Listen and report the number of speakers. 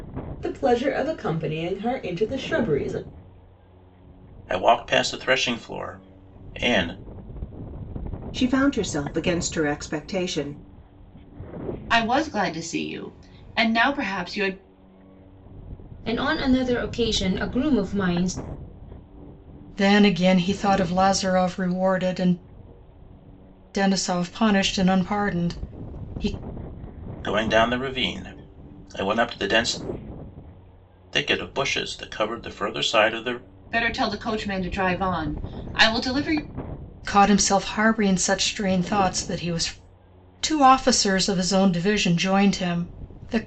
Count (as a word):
six